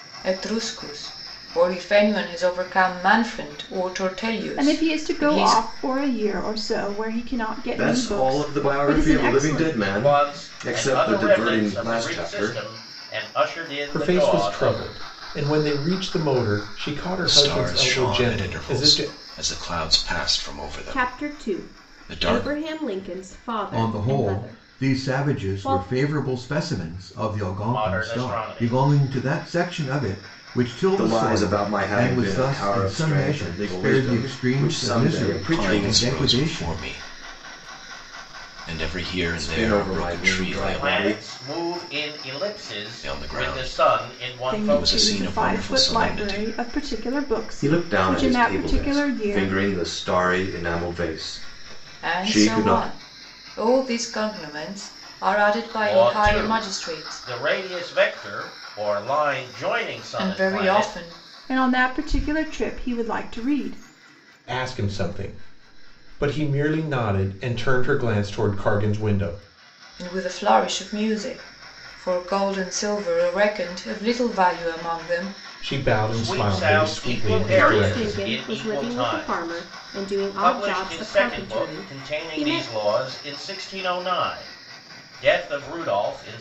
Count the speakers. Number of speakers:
8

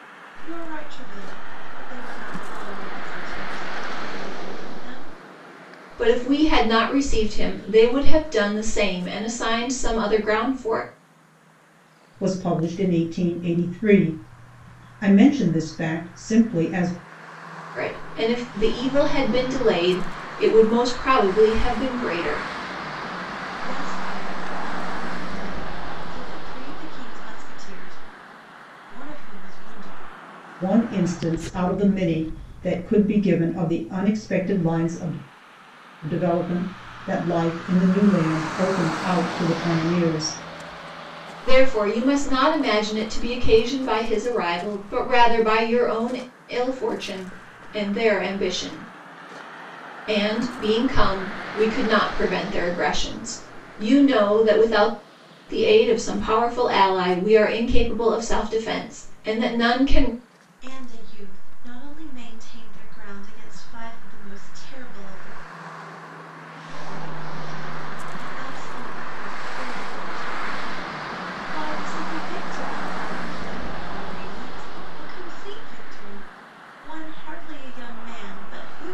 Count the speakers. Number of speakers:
3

